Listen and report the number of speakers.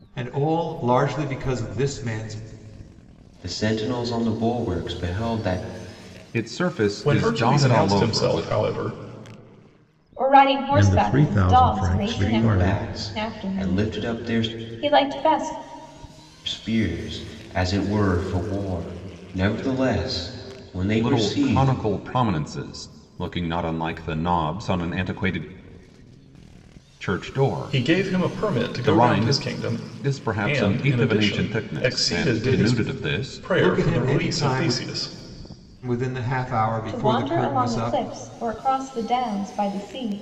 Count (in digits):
6